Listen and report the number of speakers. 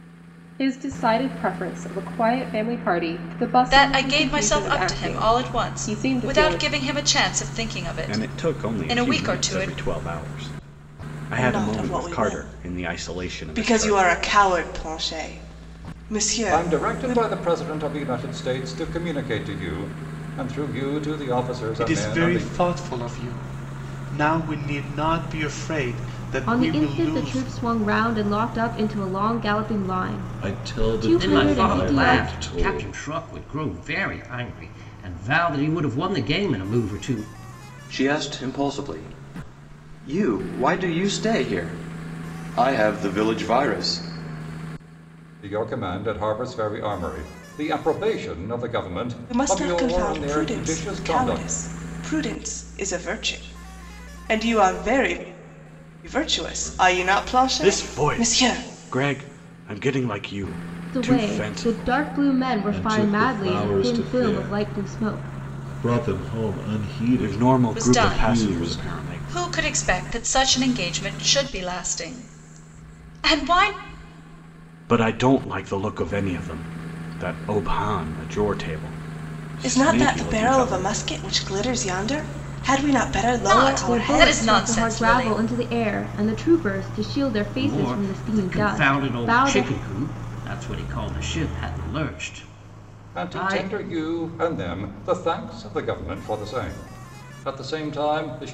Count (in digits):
10